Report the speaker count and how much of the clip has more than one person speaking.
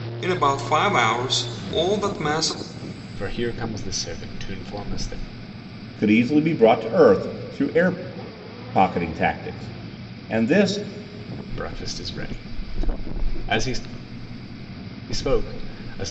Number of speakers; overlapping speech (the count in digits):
3, no overlap